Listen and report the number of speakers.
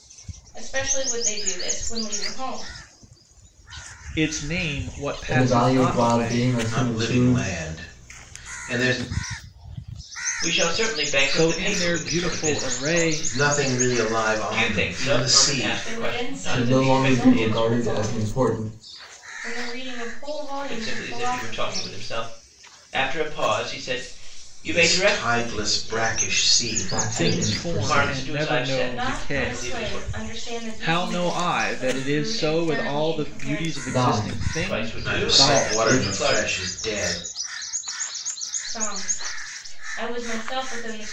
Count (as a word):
five